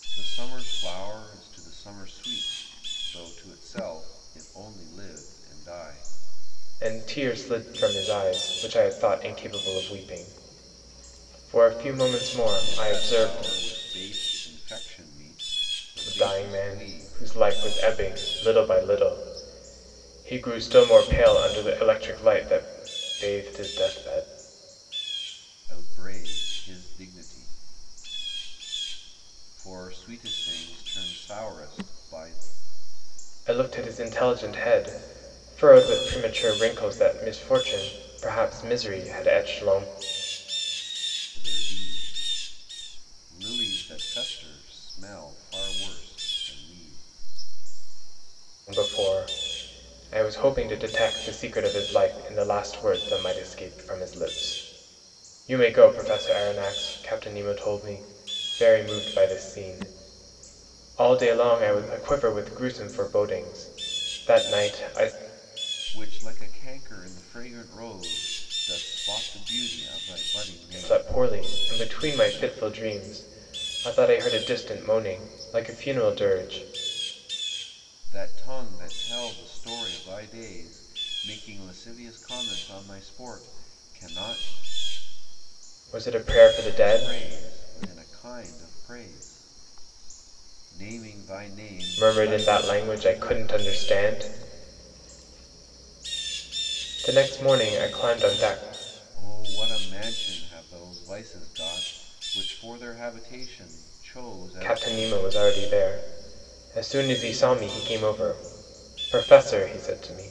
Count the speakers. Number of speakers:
2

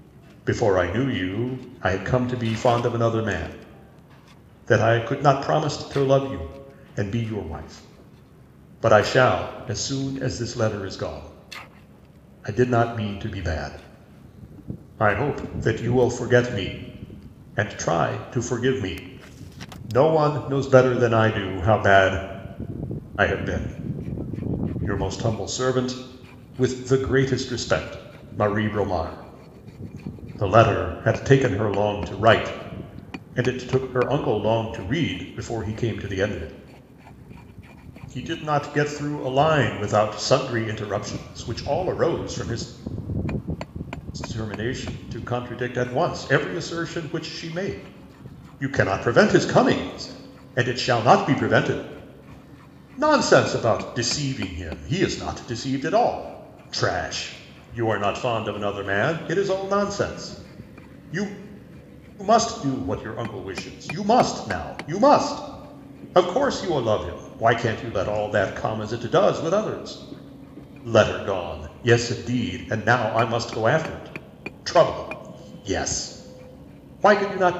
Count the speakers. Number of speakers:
1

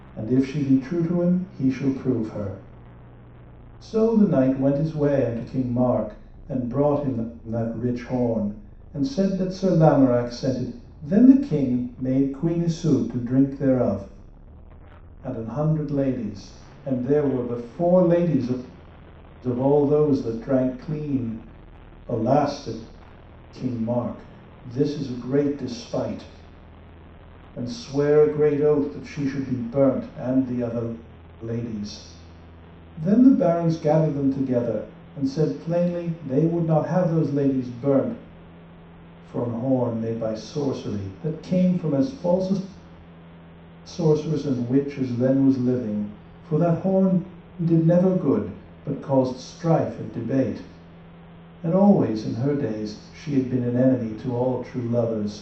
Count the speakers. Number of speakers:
1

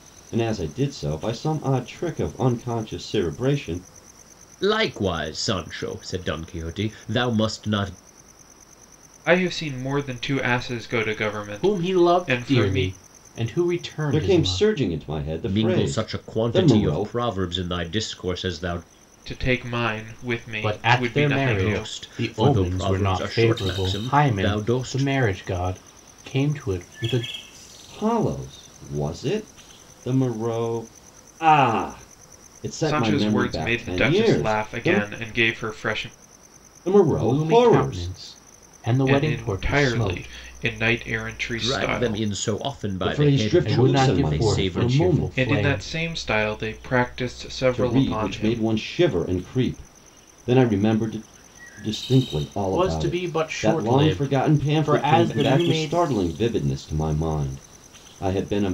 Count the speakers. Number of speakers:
4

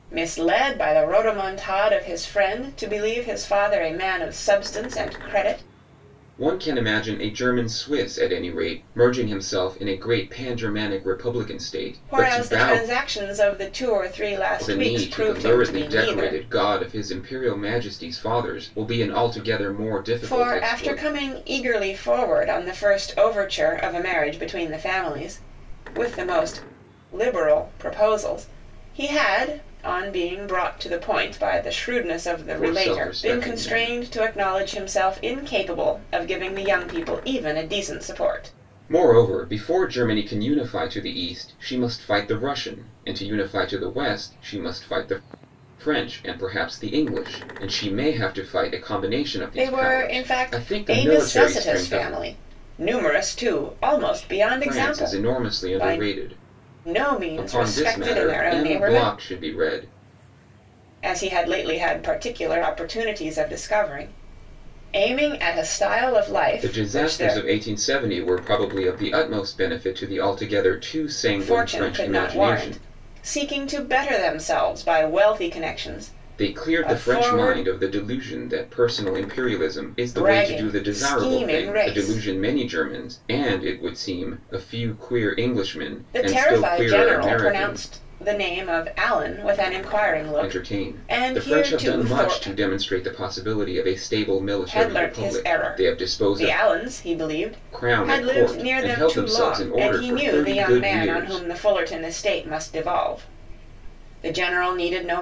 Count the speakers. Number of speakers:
2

